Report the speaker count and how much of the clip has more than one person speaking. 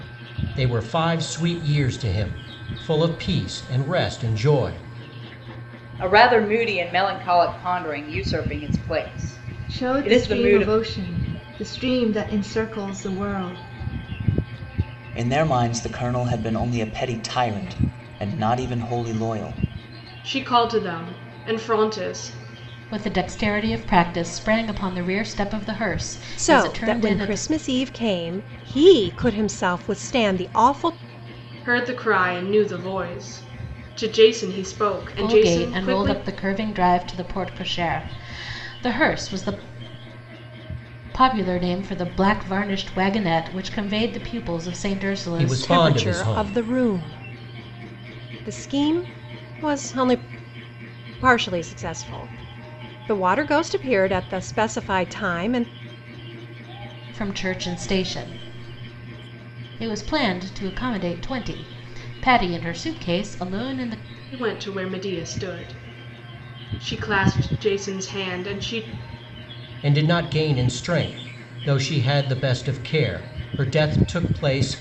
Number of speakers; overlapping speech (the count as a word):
seven, about 6%